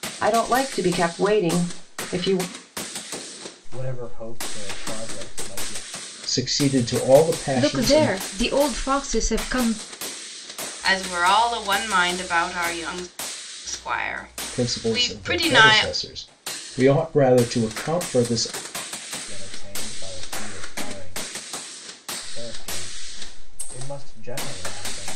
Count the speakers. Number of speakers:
five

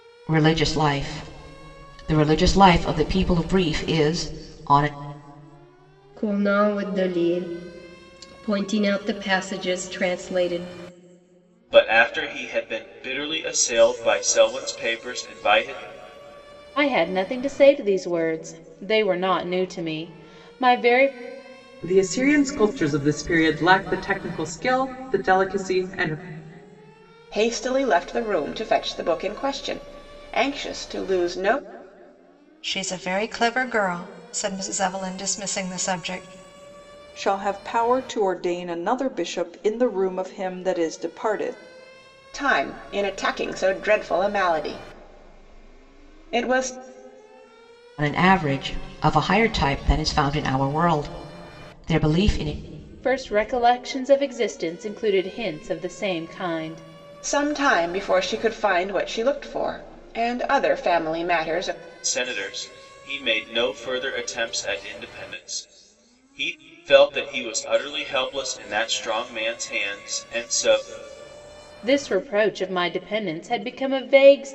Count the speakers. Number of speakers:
eight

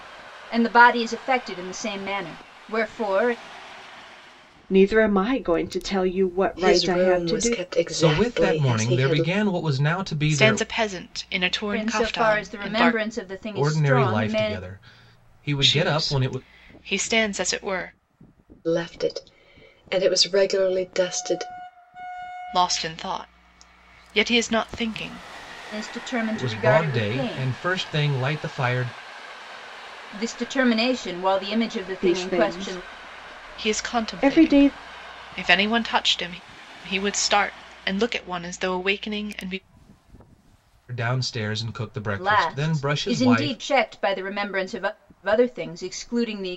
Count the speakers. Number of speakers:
five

